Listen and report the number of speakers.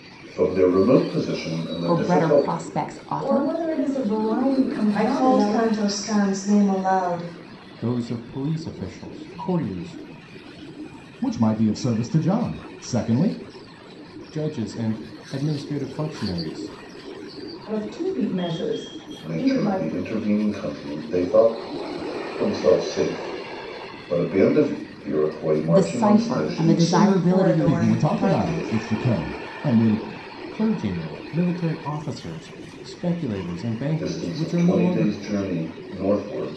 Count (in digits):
6